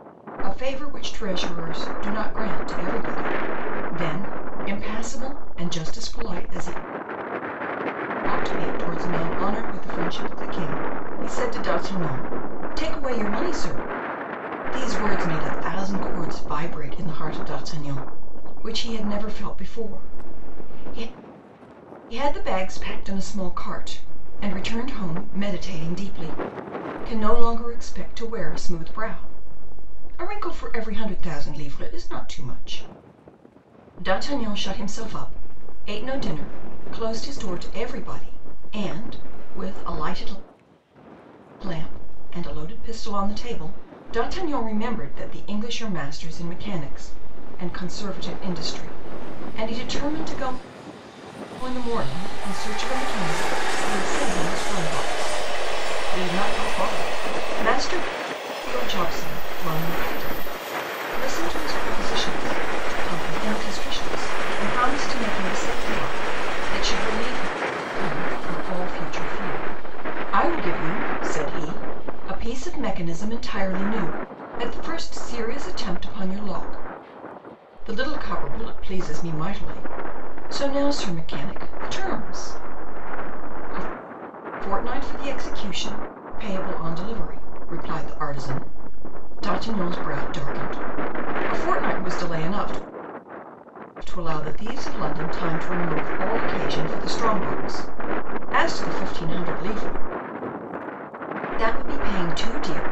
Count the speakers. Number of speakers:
one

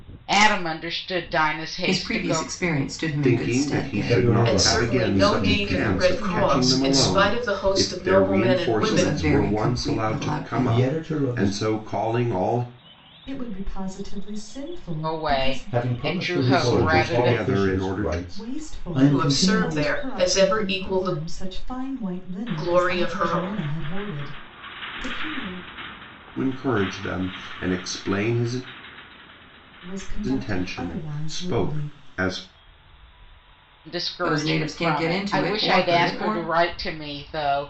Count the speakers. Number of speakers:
six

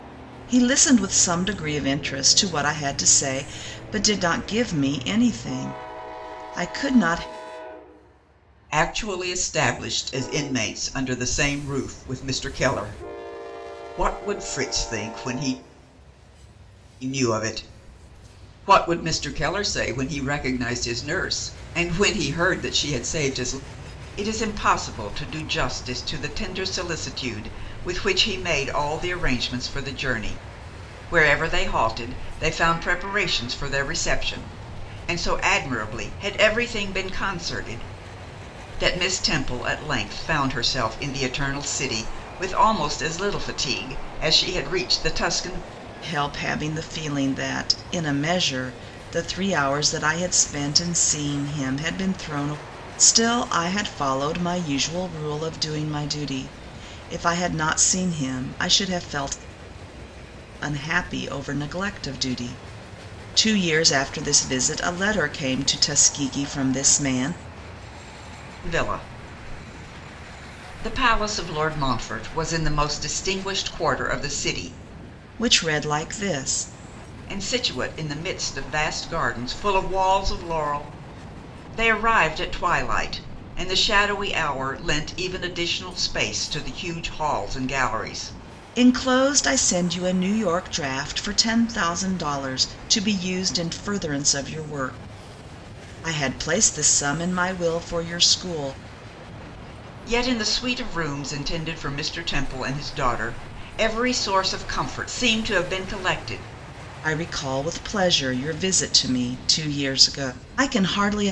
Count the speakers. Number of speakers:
two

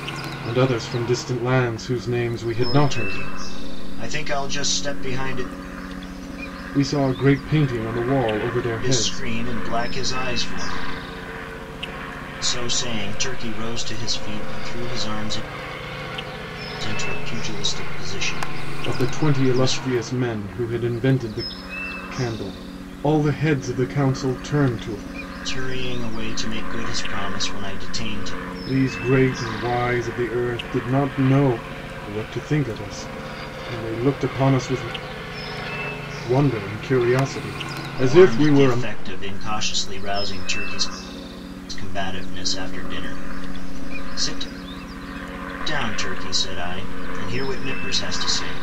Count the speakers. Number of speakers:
two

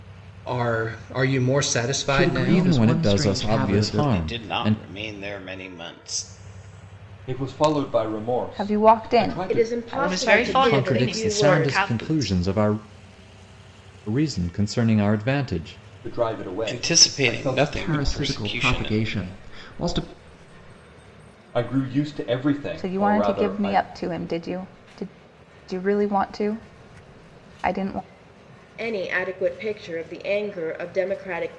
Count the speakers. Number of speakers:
eight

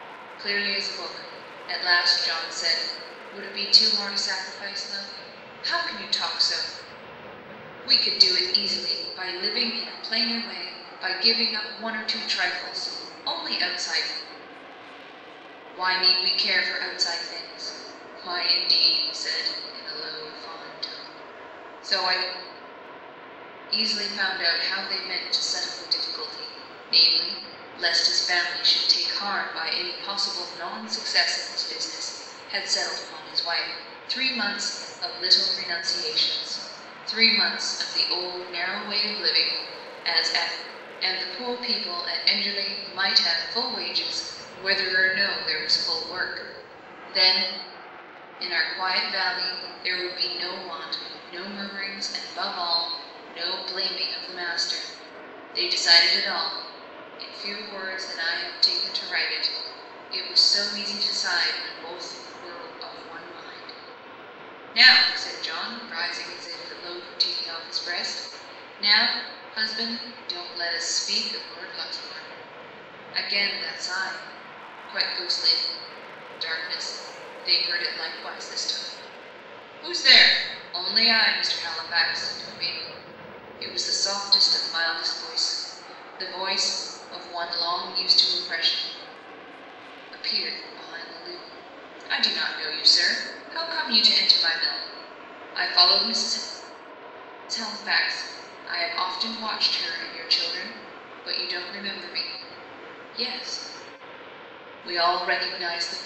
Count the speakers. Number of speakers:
one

